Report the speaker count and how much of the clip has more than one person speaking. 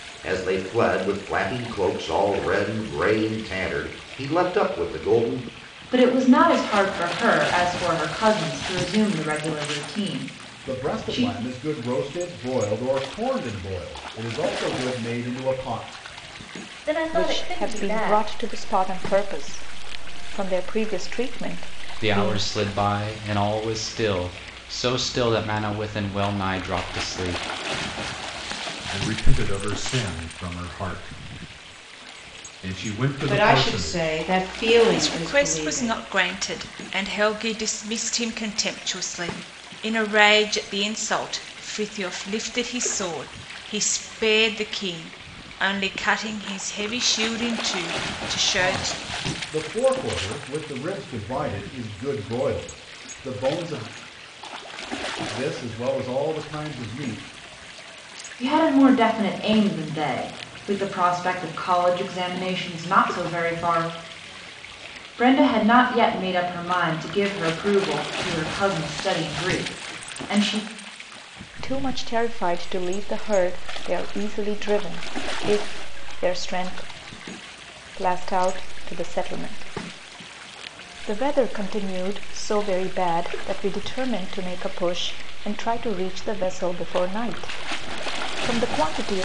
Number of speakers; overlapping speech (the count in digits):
9, about 6%